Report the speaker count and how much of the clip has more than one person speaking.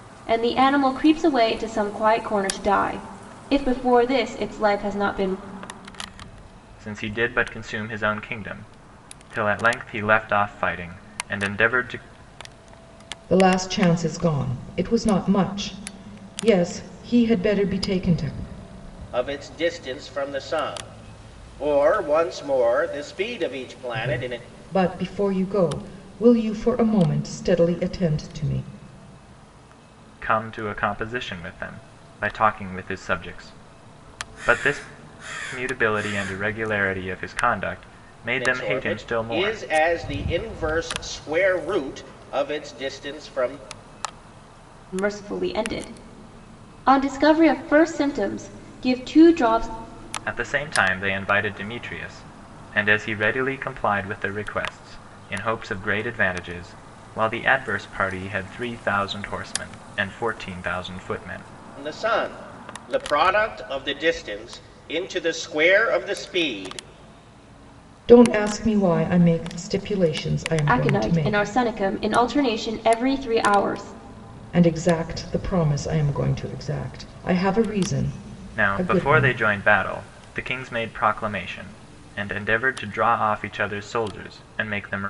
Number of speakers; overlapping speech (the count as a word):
four, about 4%